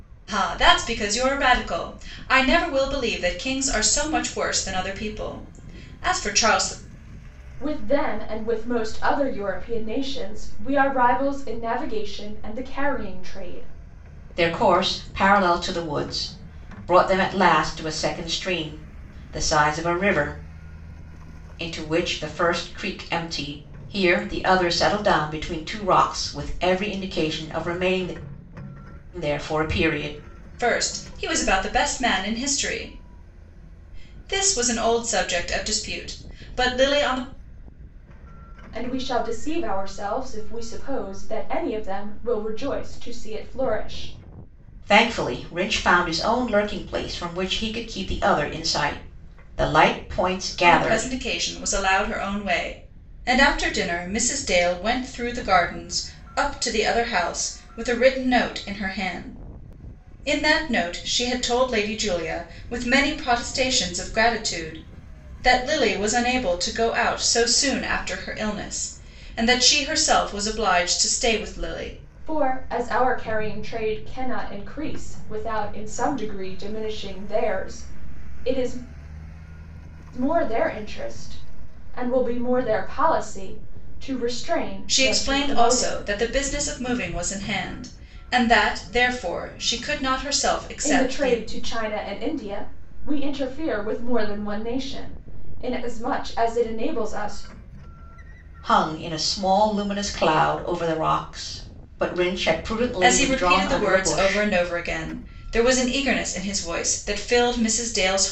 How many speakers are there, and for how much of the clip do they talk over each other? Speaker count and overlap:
three, about 3%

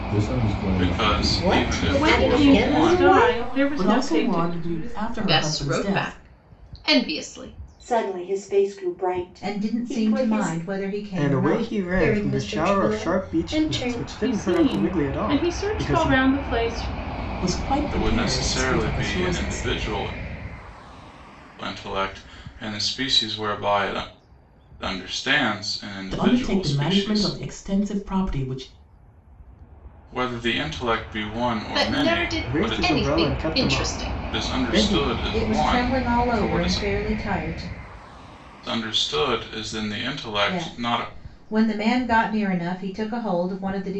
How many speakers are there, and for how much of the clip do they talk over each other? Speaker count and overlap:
ten, about 46%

